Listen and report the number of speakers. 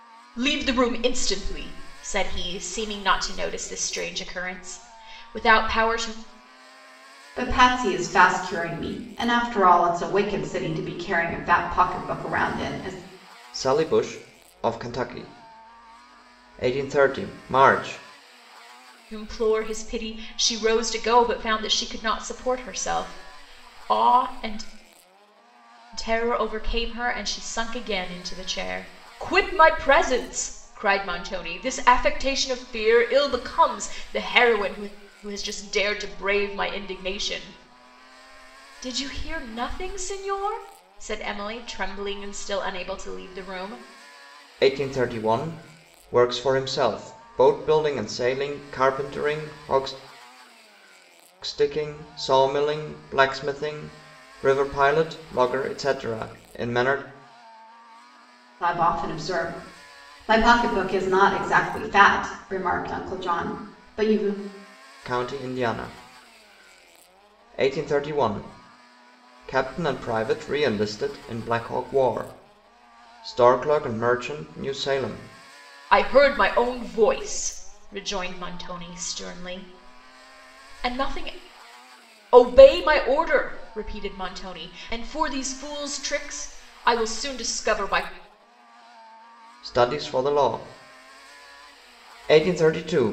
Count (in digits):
3